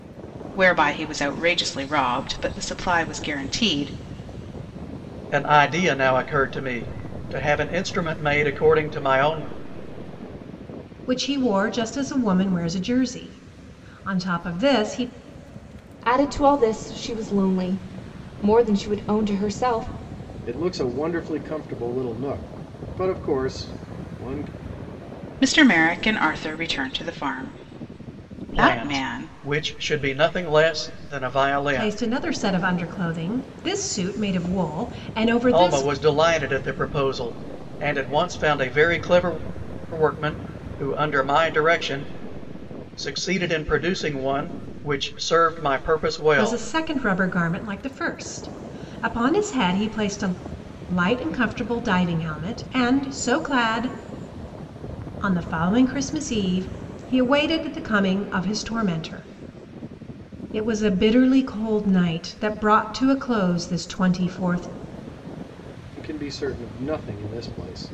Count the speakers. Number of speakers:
5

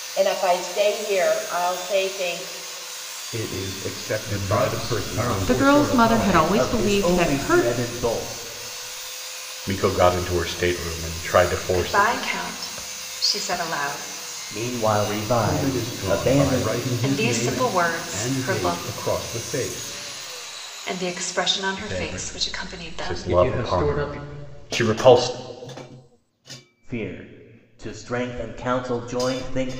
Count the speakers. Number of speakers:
7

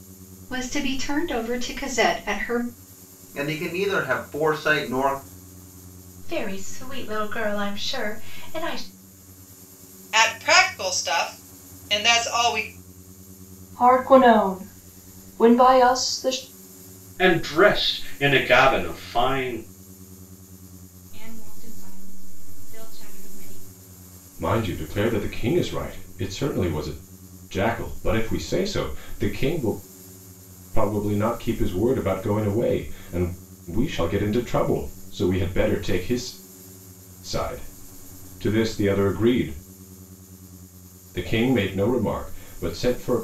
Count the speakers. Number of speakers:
8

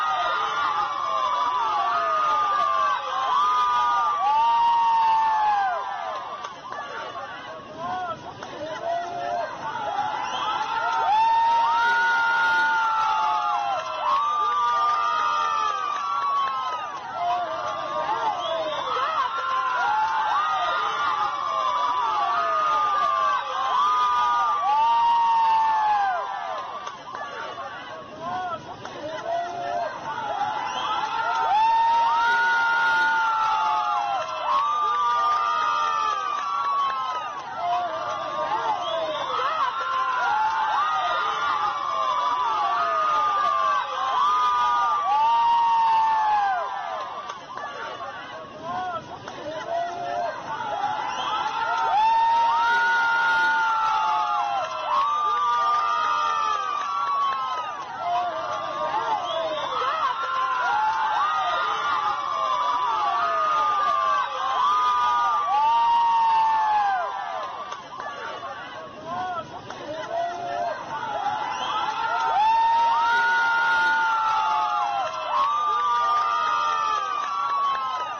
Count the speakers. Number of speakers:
0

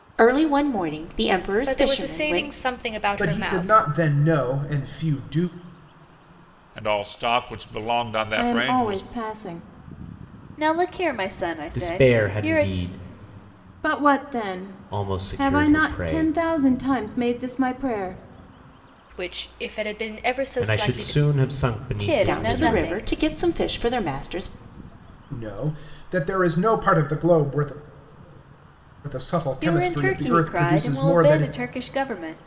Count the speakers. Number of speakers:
7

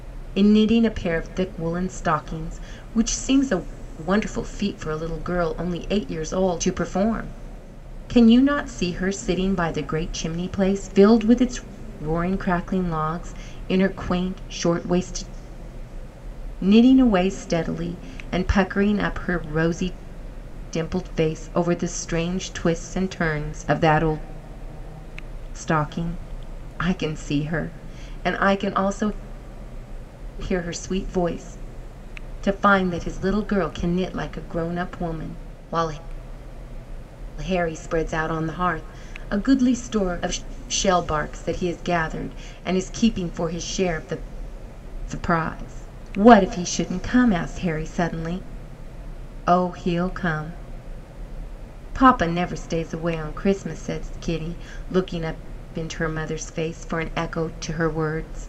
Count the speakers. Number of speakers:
1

